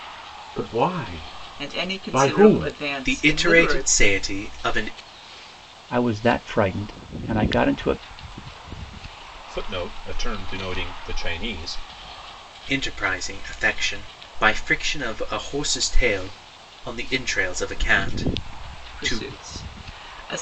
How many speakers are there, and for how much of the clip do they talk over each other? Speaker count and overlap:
5, about 12%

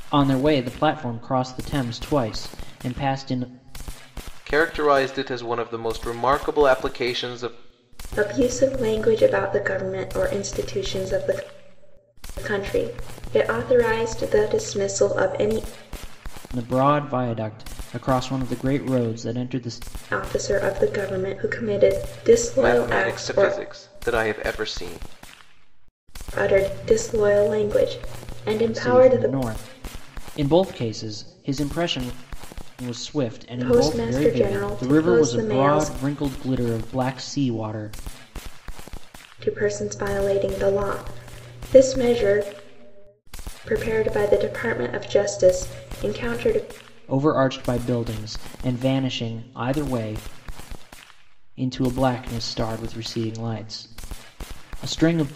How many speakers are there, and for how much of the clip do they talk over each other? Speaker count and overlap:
3, about 7%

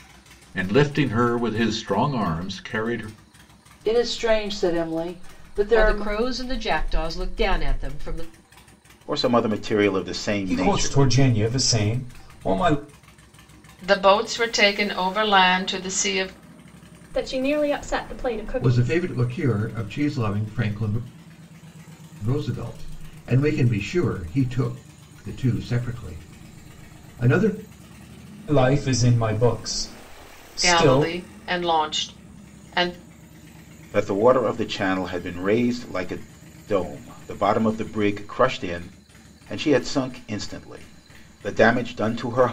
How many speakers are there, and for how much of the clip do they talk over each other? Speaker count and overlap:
8, about 5%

